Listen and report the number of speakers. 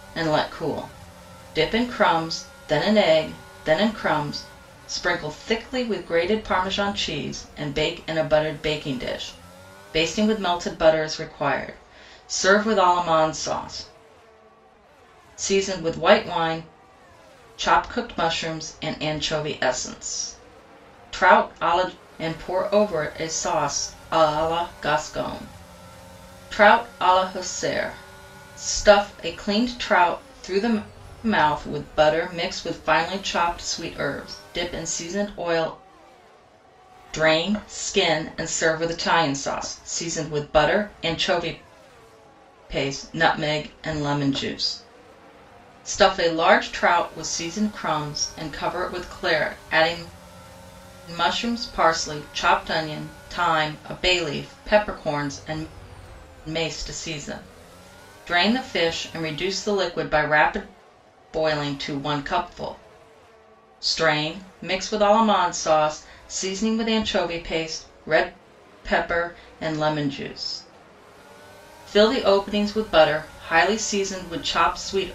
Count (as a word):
one